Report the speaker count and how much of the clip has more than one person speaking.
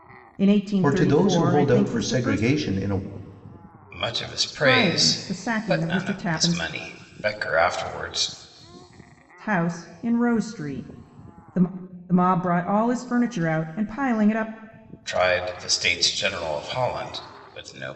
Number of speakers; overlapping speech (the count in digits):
3, about 21%